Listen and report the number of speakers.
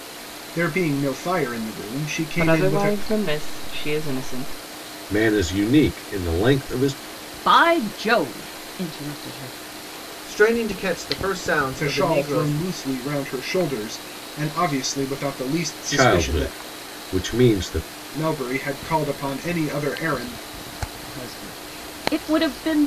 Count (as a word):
five